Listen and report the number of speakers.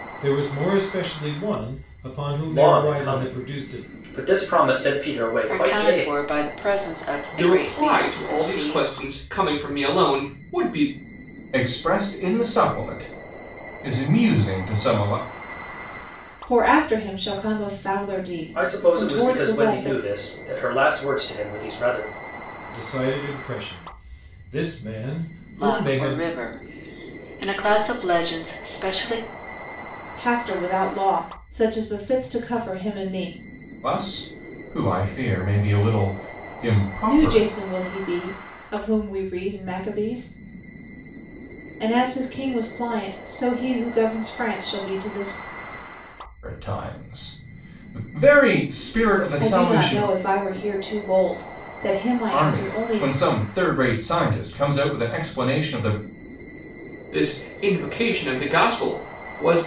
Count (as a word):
six